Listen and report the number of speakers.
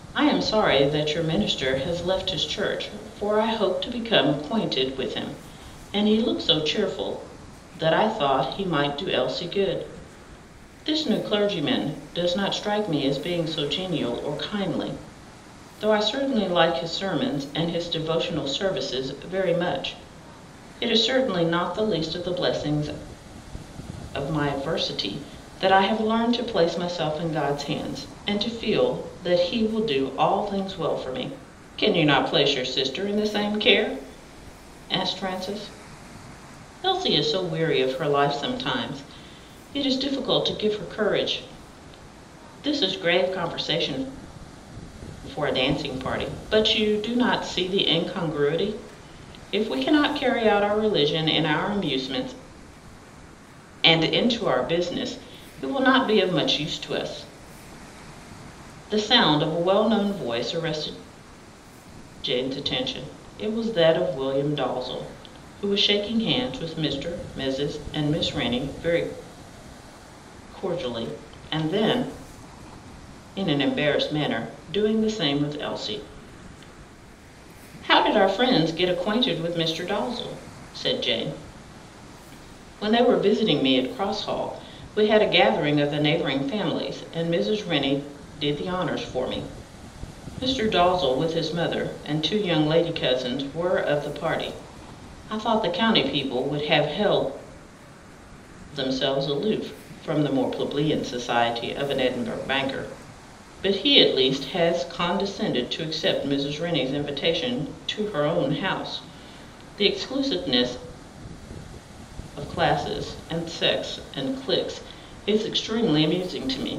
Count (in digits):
1